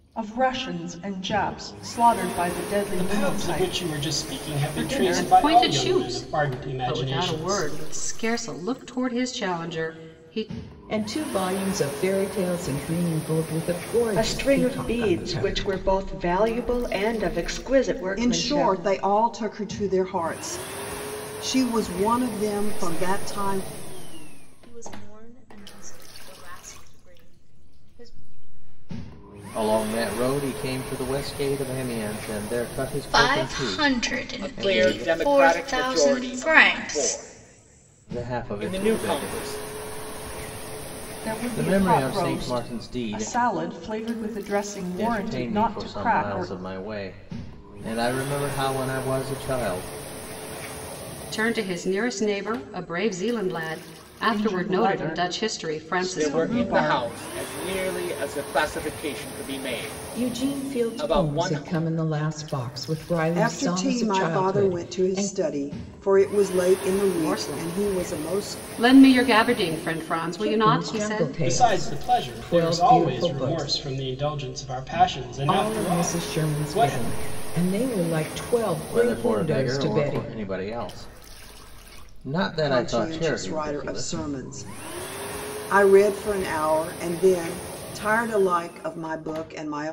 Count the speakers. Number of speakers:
ten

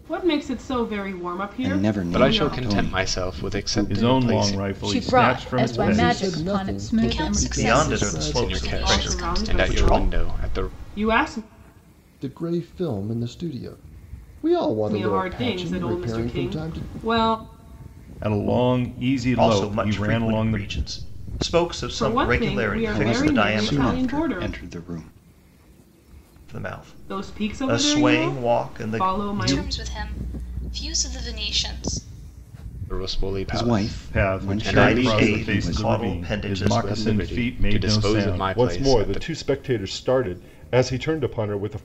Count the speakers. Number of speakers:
nine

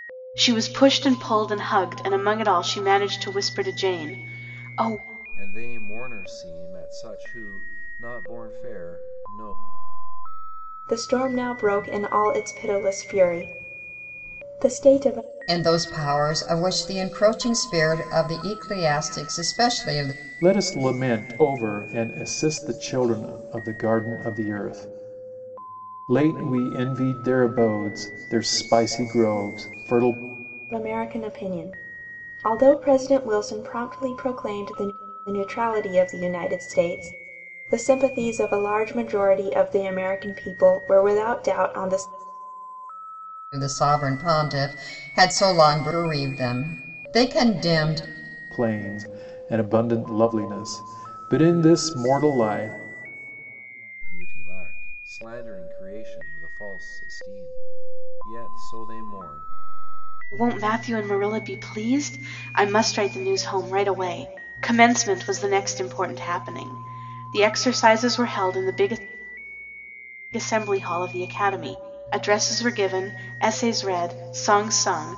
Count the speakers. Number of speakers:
five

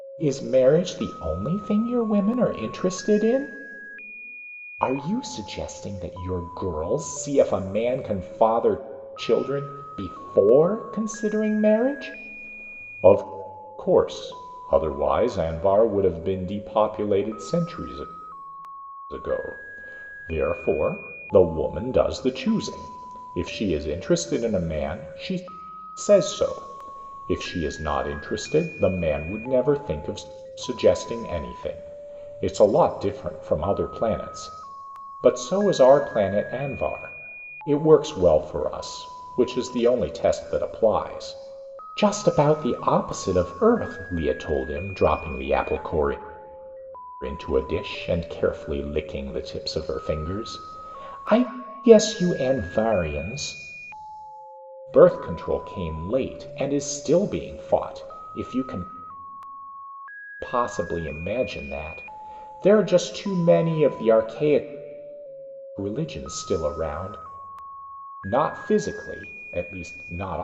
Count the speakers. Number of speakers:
one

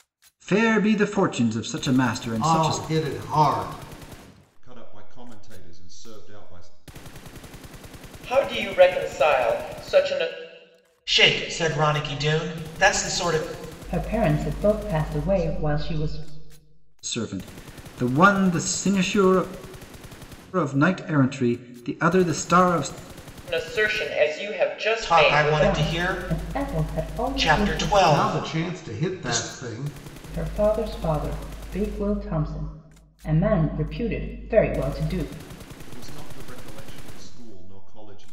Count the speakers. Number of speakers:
six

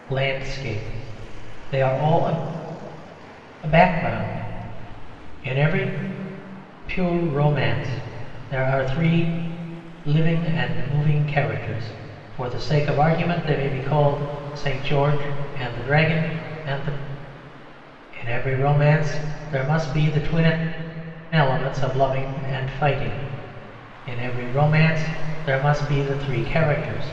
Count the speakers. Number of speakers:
one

